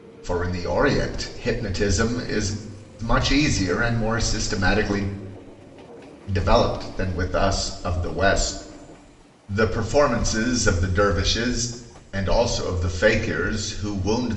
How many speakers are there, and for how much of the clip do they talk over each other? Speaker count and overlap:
1, no overlap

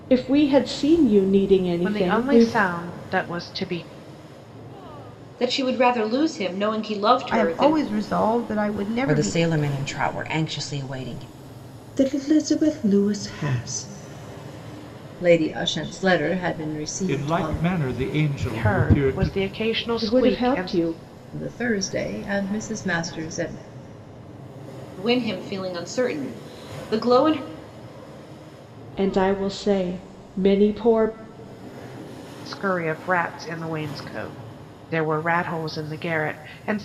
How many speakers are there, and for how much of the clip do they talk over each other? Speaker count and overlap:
8, about 10%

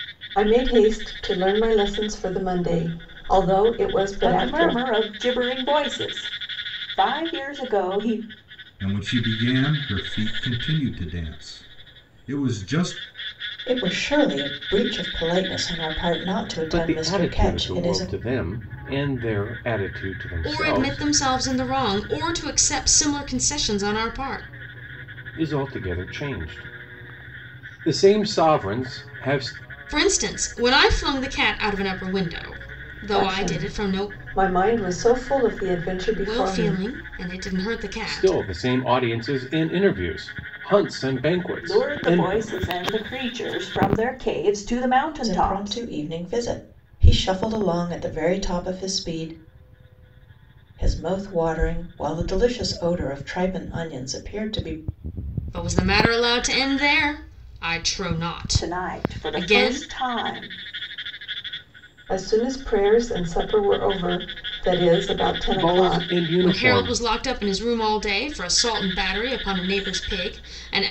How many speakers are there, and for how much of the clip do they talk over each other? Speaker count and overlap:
6, about 12%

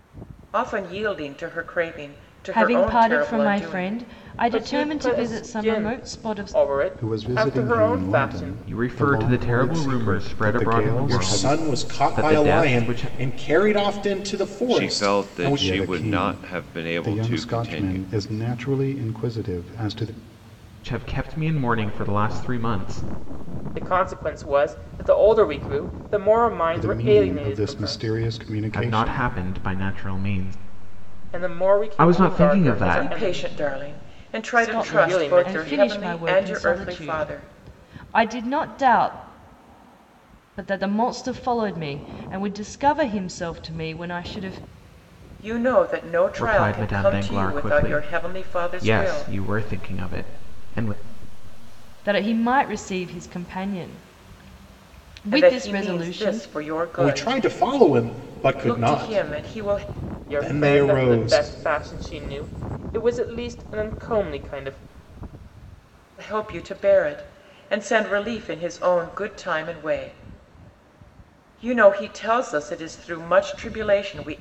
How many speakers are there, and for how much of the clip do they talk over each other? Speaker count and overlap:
7, about 40%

